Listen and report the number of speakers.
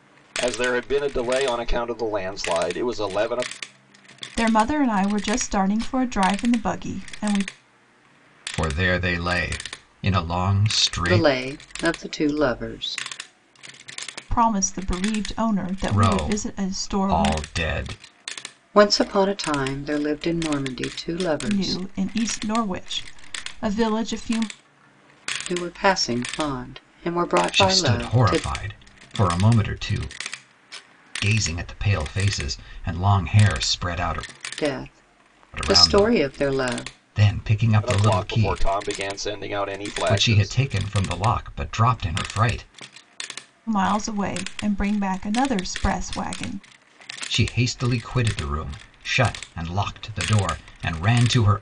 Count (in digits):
4